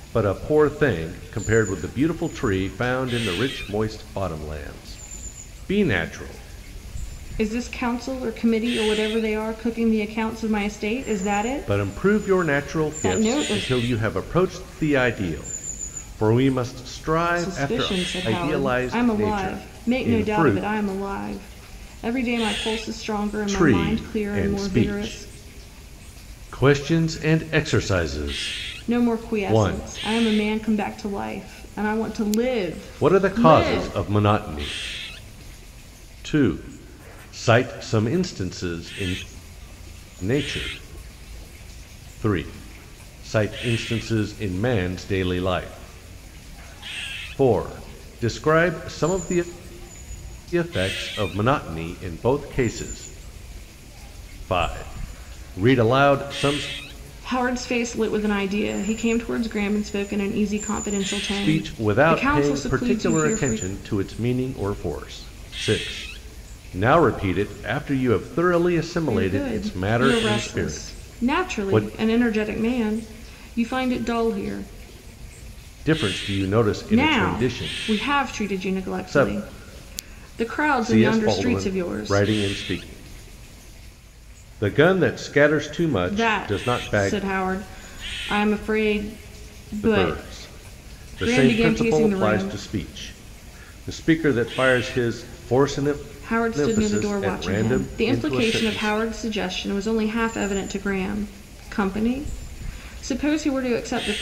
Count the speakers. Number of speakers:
2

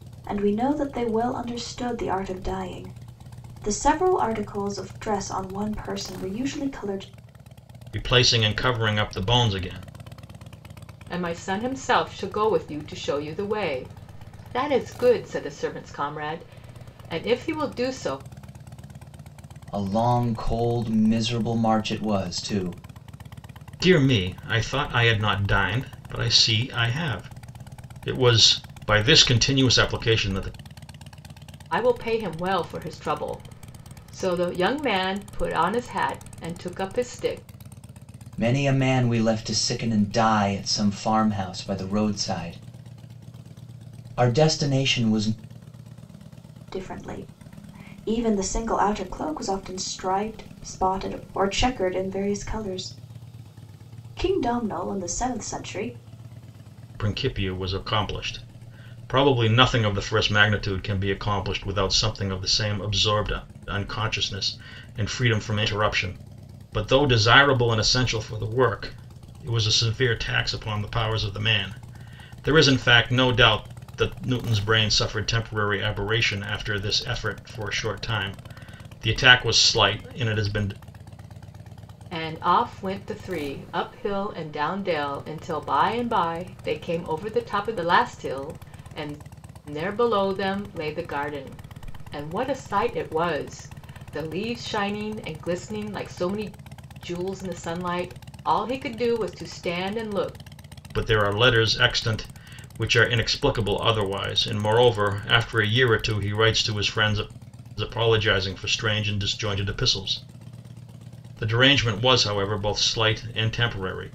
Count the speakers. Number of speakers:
4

